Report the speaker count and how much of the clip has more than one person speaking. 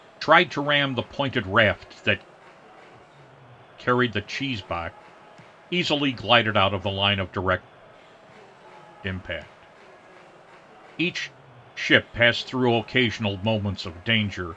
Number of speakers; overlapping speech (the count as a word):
one, no overlap